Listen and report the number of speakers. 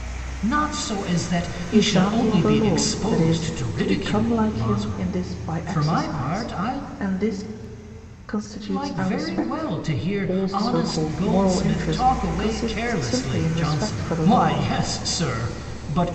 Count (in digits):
2